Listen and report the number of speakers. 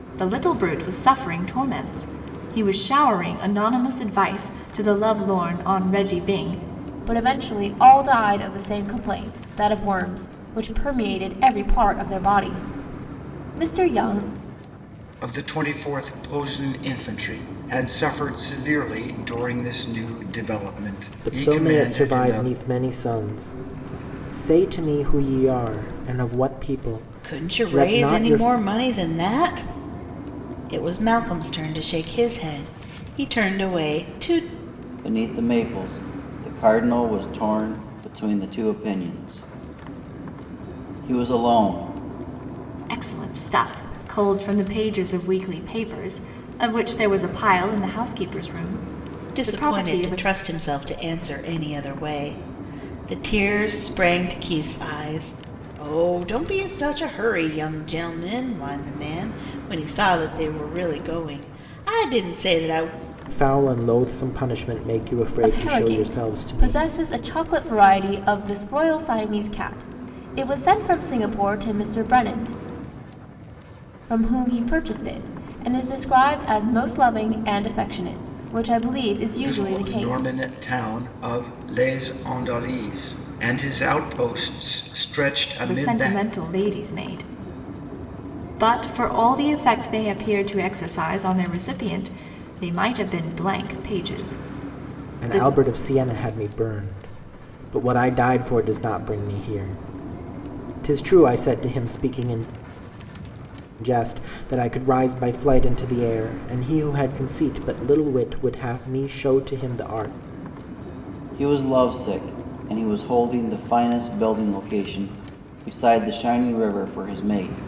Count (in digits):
6